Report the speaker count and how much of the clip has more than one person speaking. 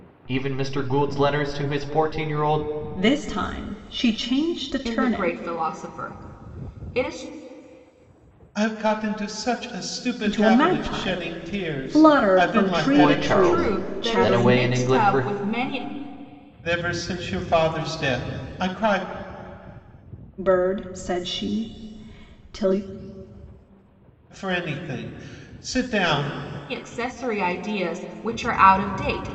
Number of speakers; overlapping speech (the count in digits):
4, about 19%